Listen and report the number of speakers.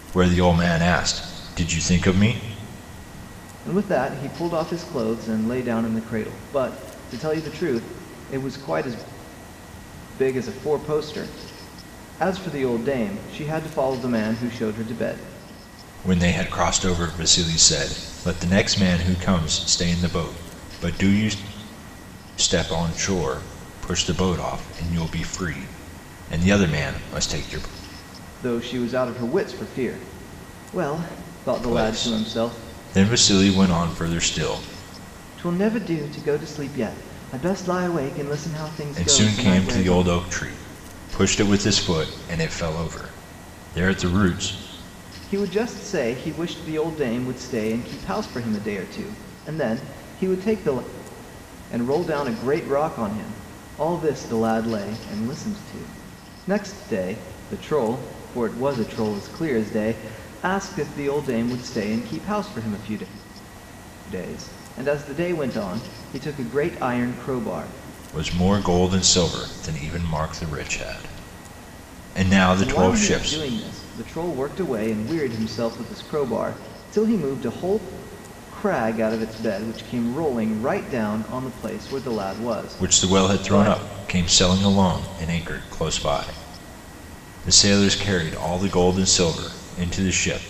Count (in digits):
2